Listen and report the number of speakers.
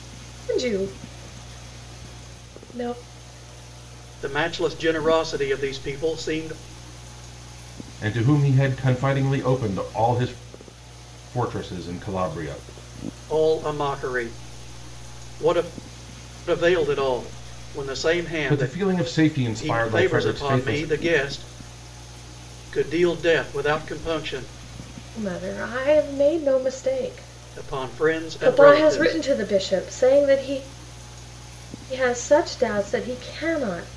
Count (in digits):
3